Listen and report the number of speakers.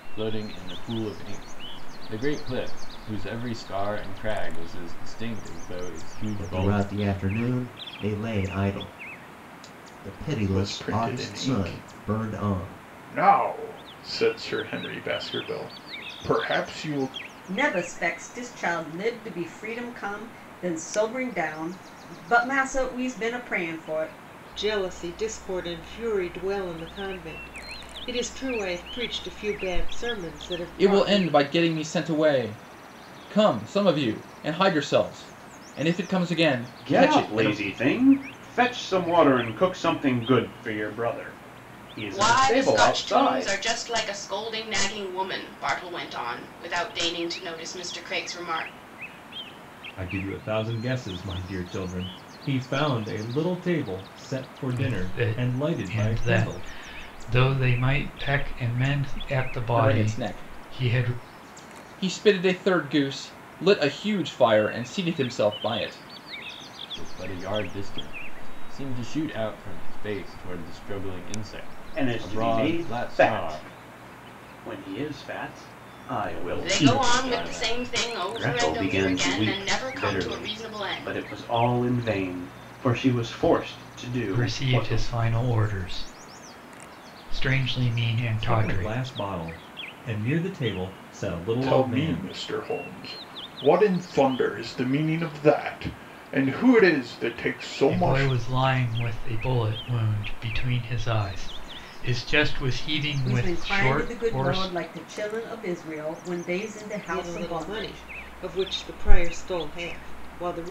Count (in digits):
10